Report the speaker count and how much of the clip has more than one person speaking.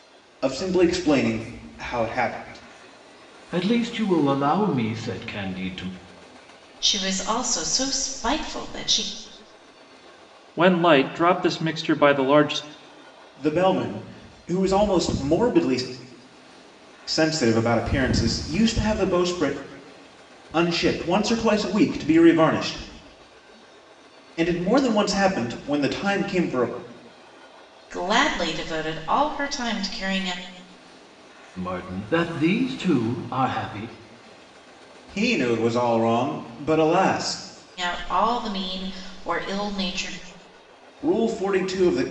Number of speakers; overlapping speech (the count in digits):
4, no overlap